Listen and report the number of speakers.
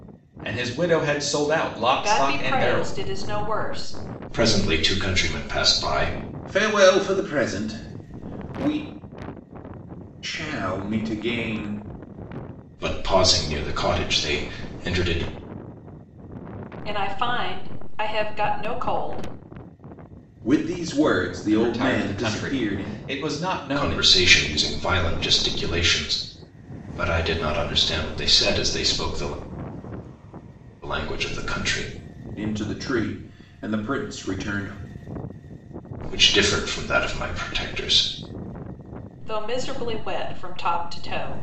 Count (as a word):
four